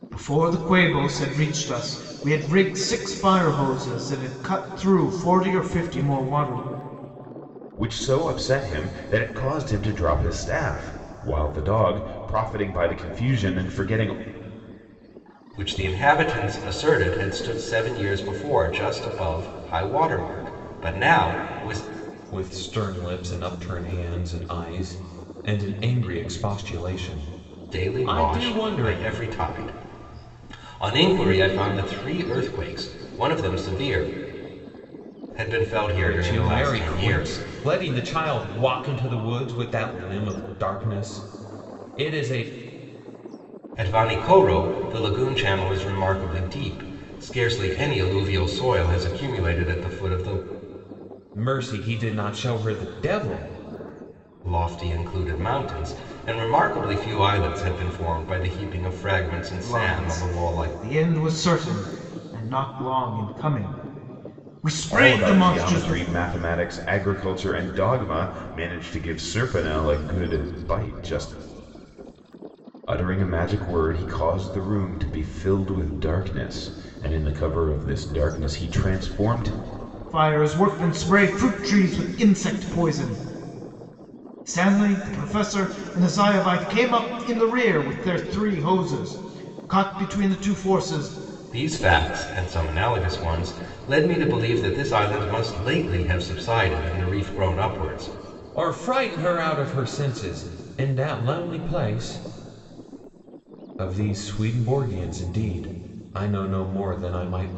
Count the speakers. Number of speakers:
4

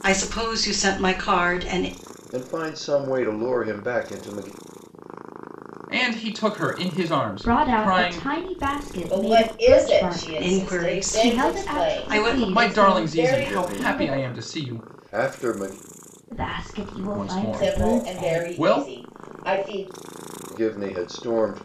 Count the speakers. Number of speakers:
5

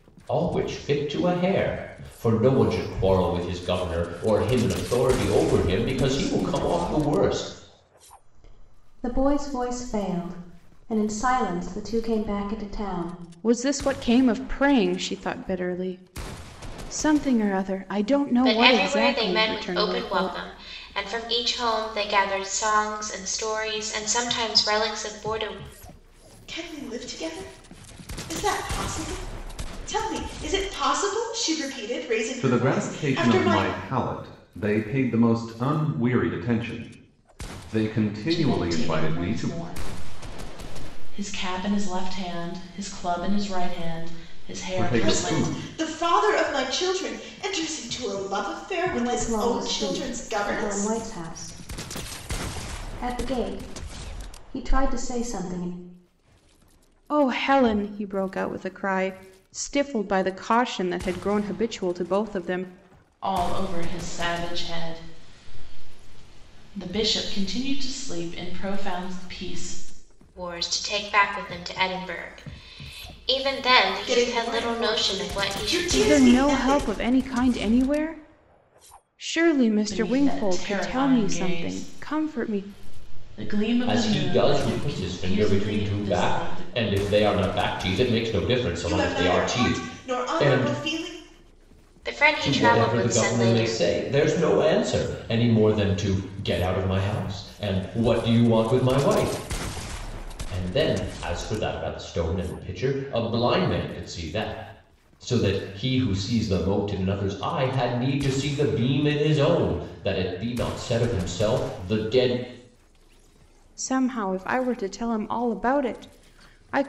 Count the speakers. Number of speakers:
7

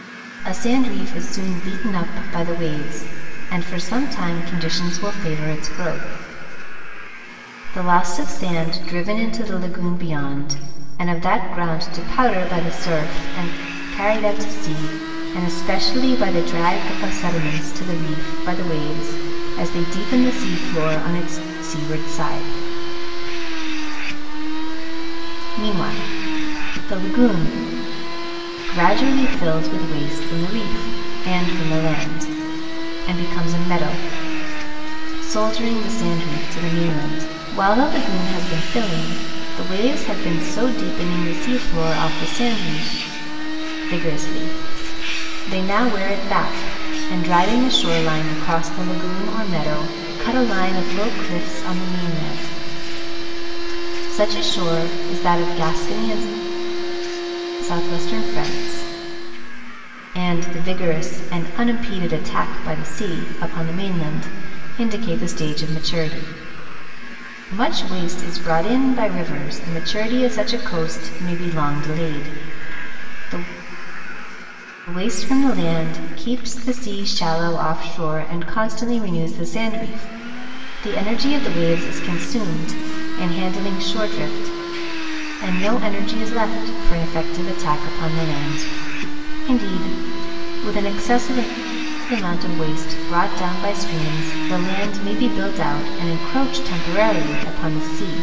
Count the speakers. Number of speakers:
1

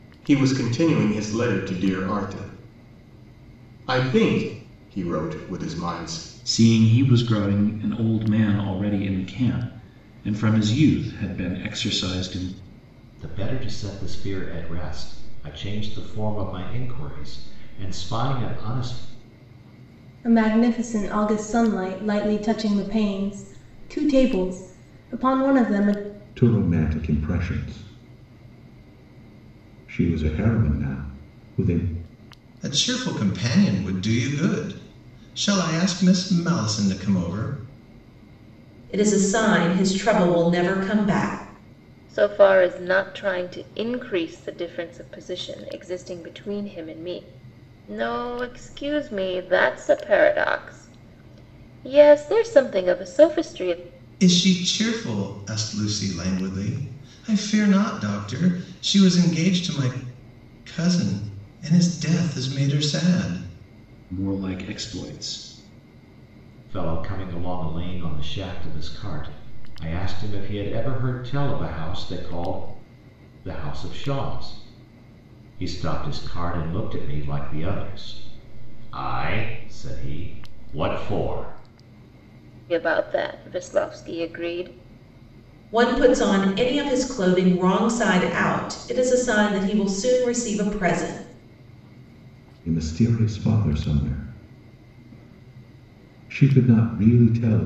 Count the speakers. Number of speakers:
8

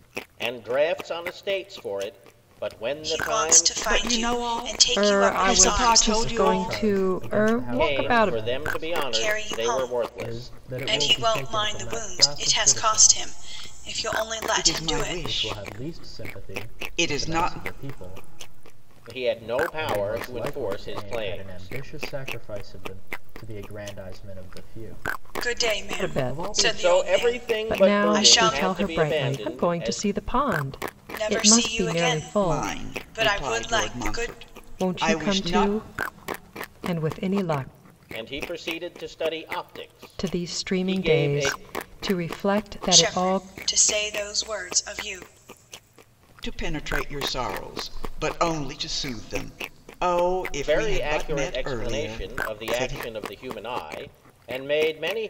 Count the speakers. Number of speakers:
5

